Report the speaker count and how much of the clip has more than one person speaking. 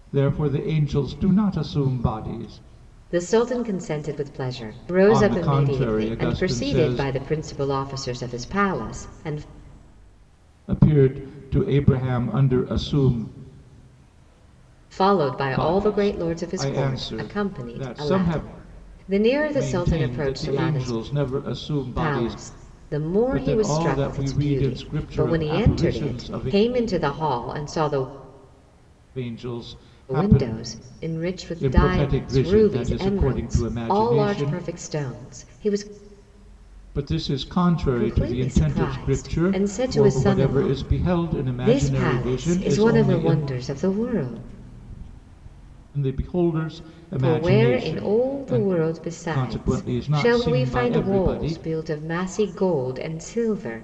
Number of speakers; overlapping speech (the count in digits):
2, about 42%